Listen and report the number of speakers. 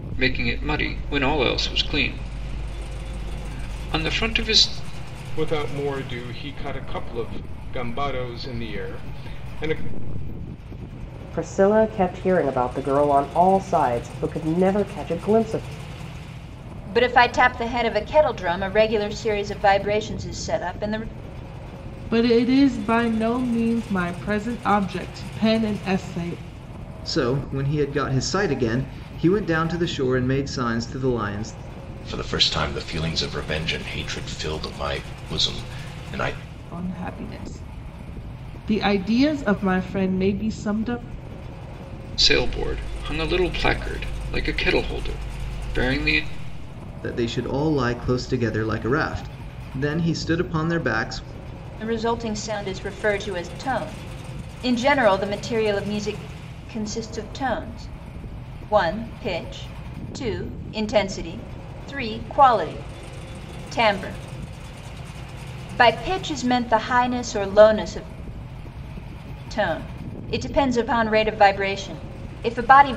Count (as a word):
seven